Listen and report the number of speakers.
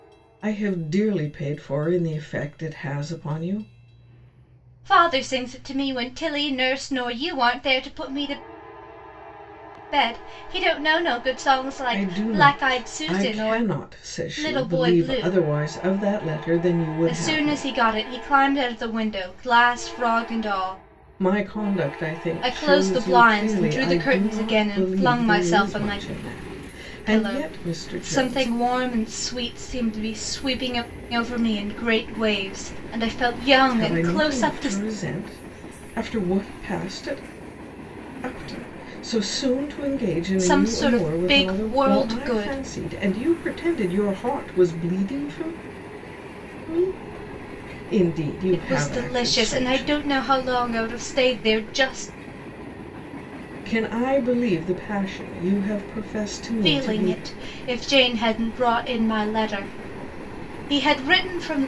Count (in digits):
2